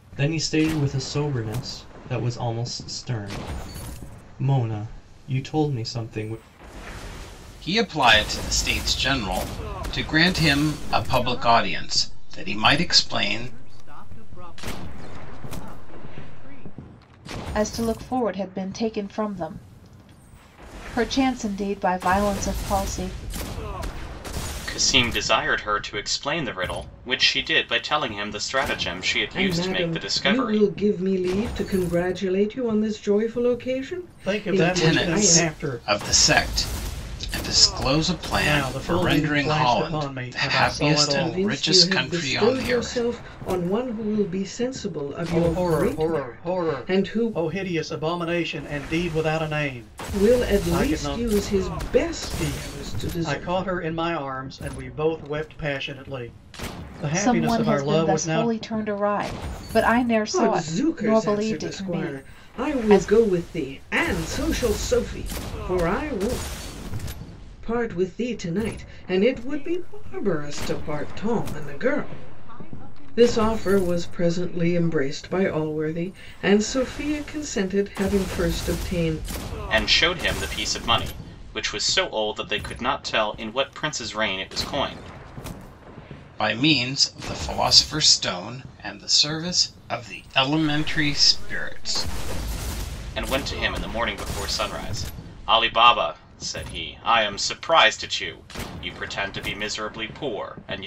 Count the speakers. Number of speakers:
seven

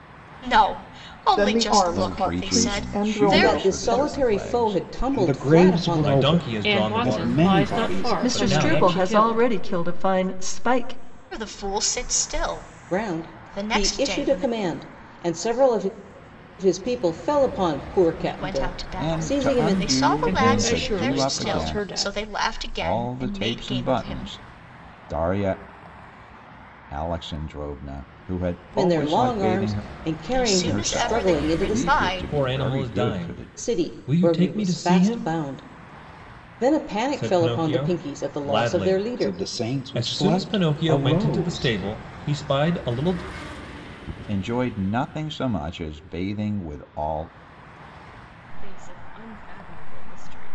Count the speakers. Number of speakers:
nine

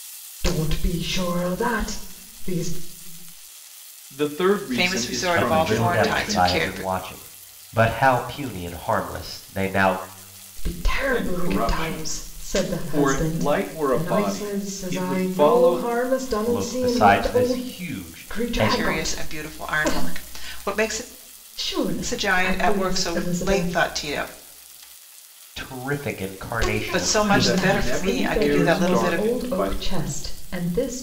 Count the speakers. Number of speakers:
four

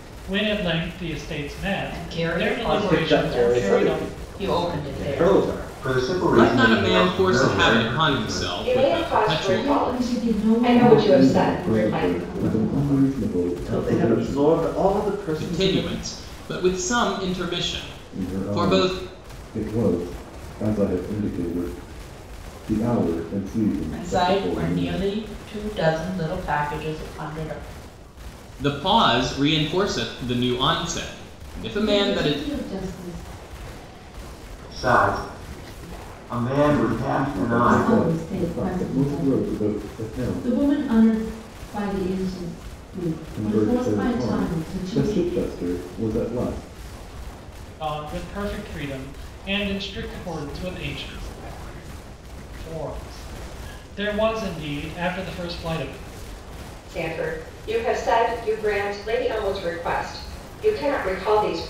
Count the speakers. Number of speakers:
eight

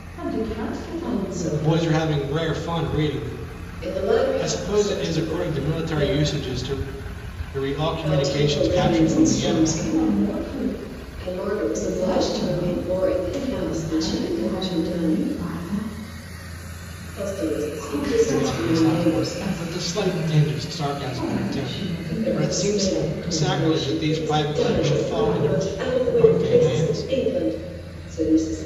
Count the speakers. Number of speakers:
three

